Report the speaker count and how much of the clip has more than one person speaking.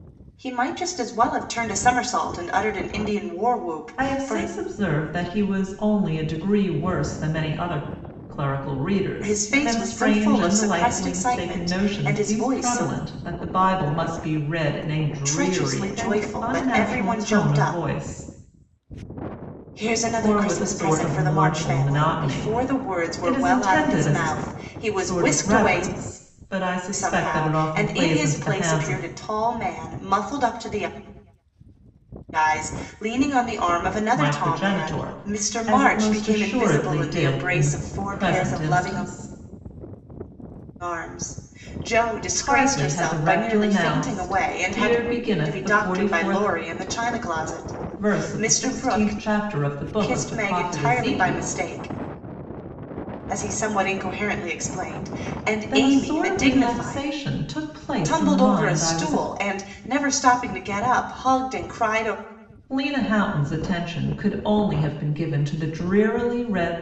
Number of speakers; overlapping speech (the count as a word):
two, about 42%